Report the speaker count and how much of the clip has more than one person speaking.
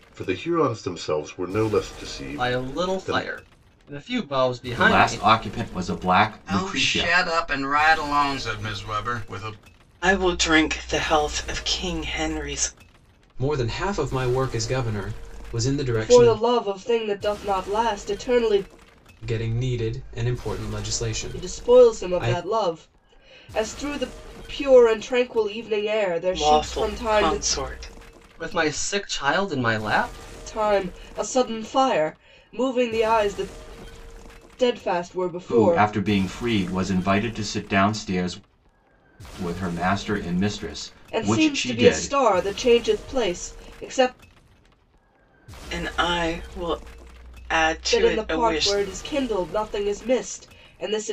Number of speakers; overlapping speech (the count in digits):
7, about 15%